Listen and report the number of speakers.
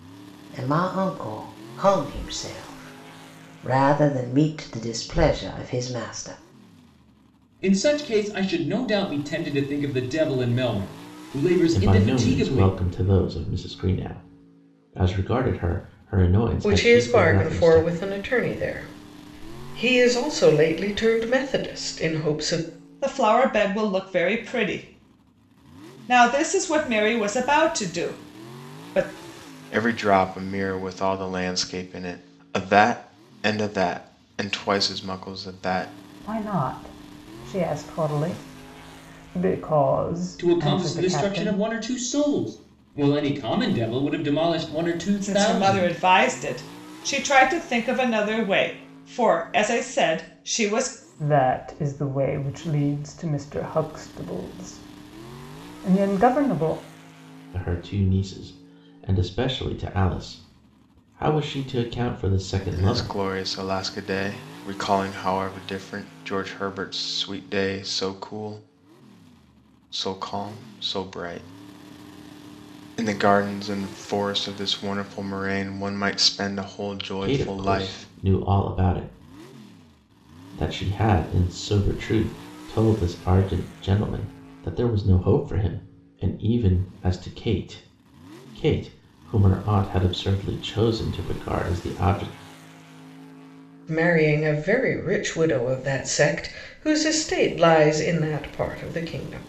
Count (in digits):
7